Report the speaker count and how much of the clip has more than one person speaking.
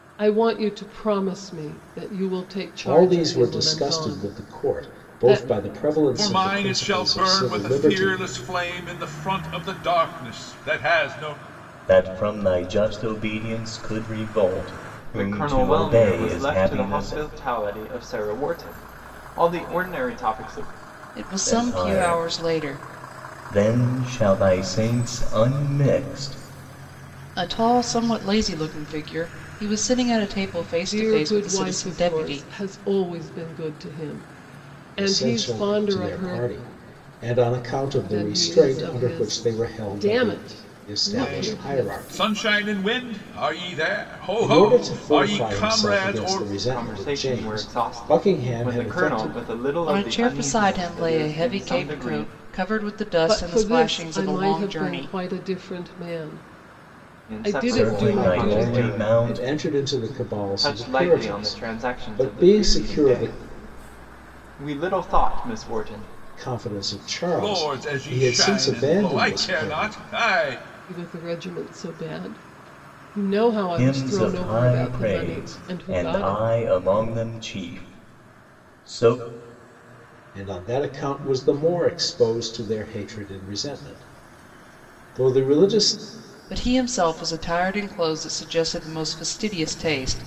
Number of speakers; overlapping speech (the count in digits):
6, about 39%